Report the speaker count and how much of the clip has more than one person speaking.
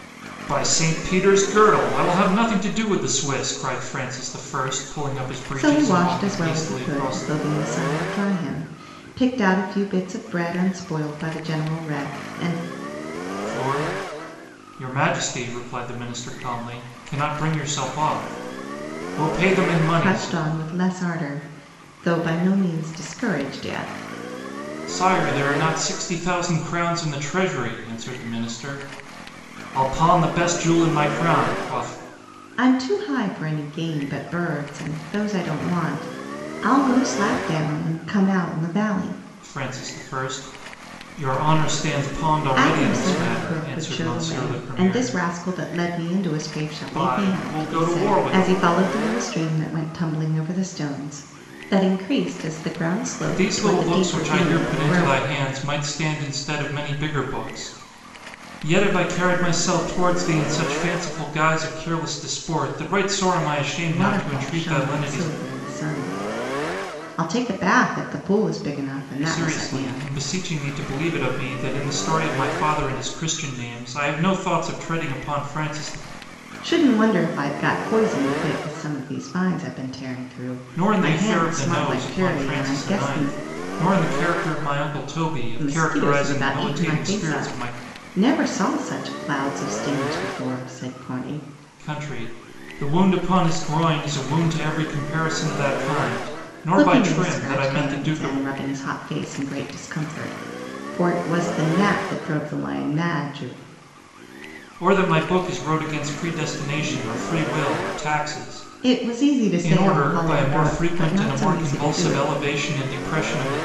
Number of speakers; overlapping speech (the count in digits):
2, about 19%